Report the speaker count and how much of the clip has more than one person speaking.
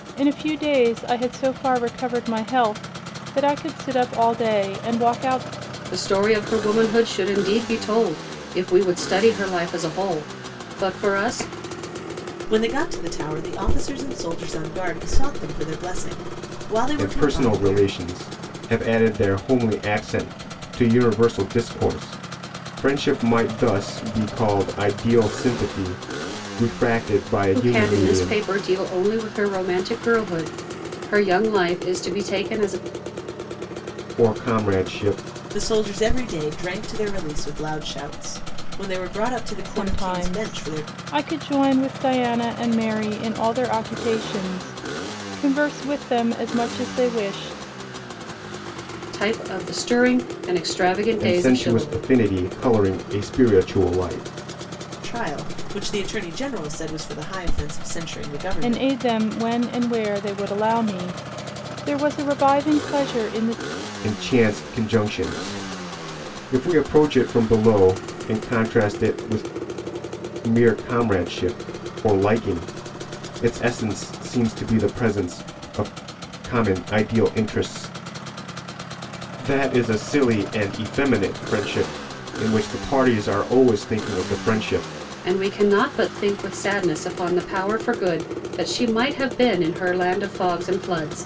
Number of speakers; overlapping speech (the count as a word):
four, about 5%